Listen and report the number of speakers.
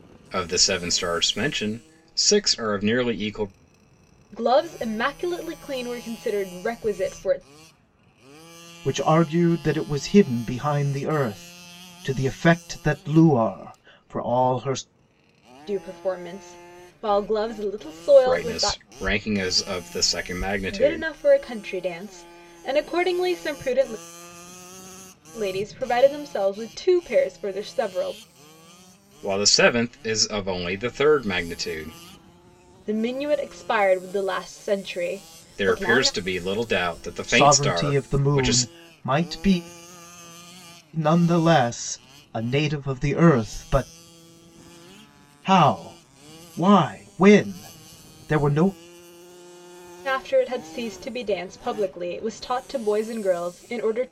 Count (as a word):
three